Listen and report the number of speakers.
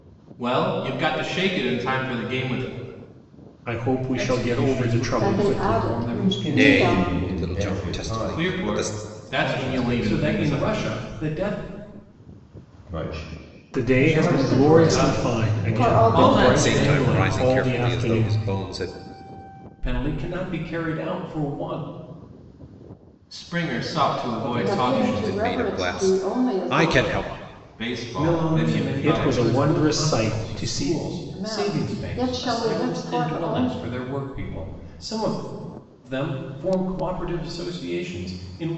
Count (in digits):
6